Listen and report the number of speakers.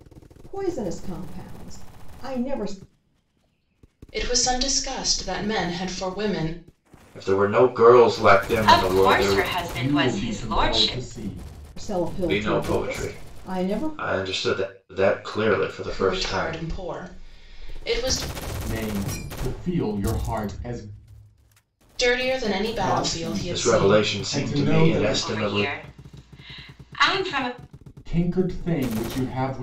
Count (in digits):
5